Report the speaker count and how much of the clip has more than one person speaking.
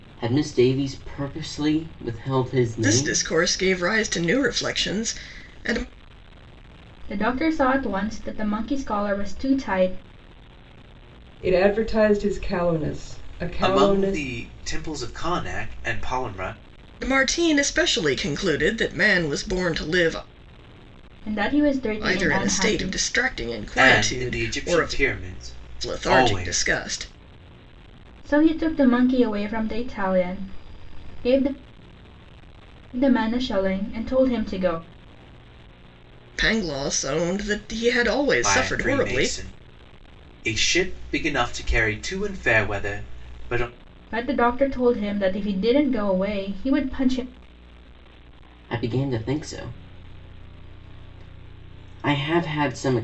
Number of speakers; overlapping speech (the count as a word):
five, about 10%